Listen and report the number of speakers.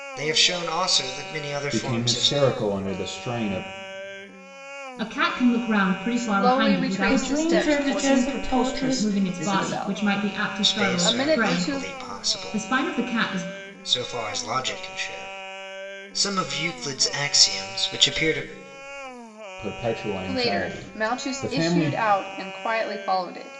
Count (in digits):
6